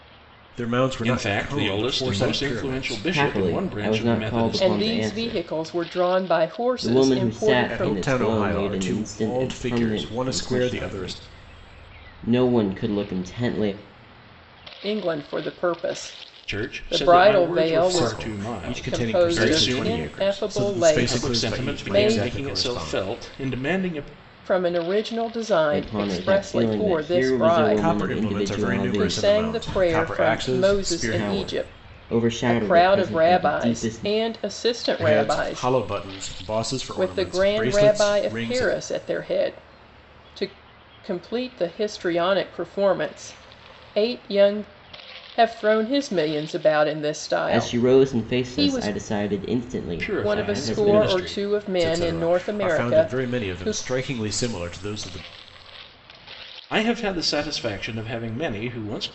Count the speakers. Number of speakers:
four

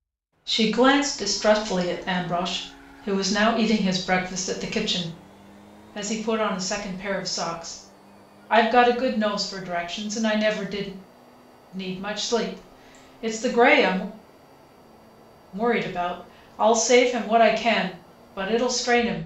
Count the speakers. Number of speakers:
one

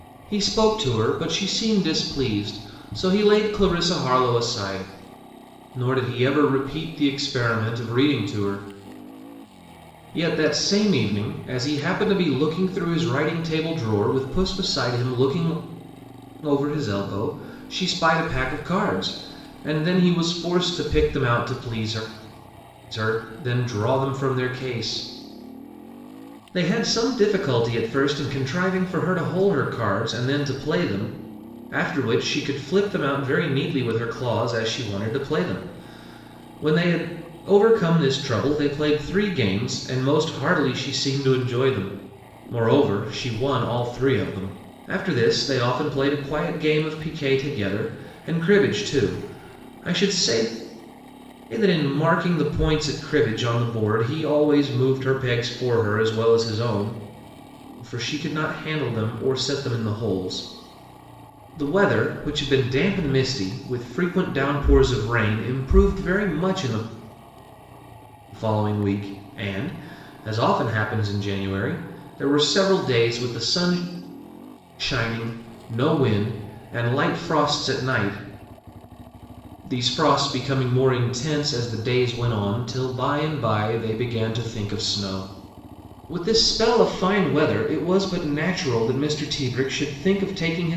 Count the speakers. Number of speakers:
one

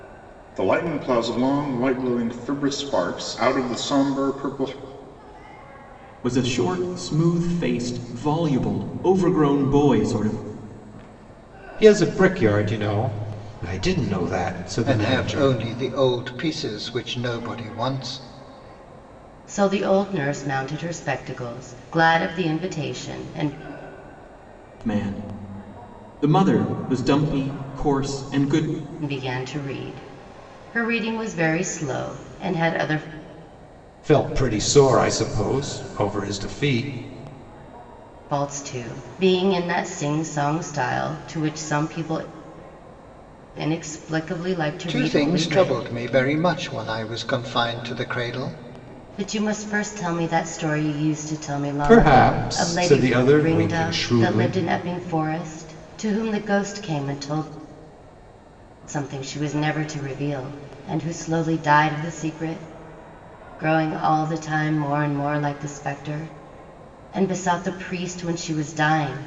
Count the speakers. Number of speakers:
five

